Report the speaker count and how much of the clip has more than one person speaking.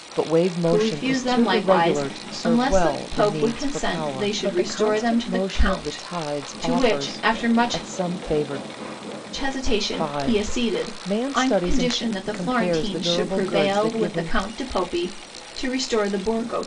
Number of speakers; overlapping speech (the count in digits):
2, about 68%